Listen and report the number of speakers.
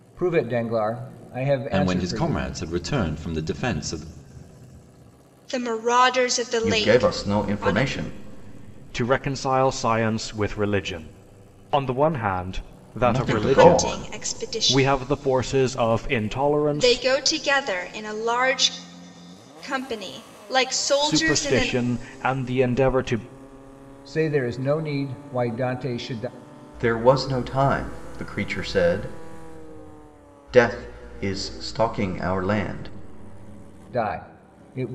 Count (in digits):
5